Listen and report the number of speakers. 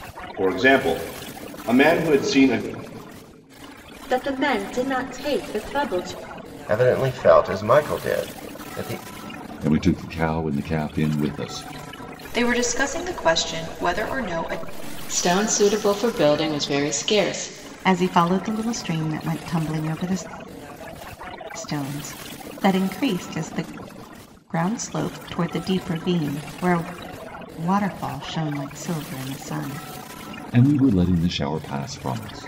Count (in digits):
7